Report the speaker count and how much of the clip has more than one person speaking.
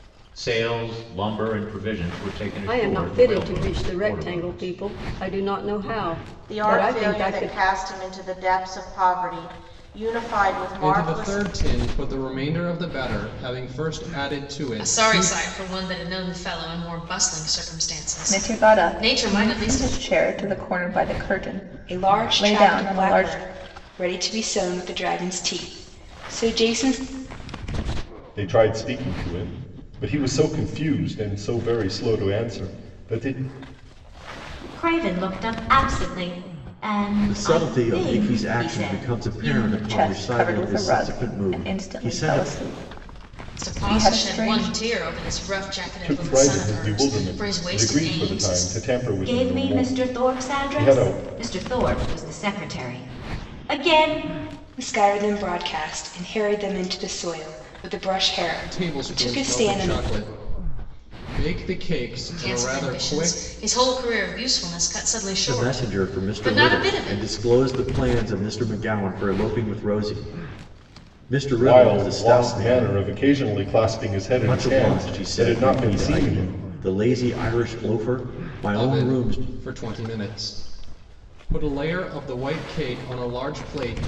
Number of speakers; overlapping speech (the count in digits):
10, about 32%